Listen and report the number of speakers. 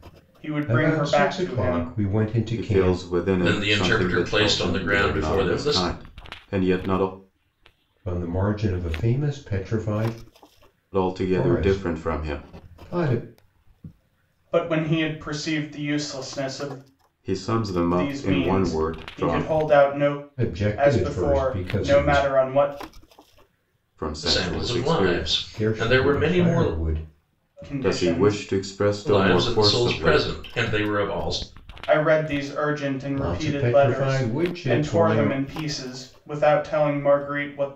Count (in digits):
4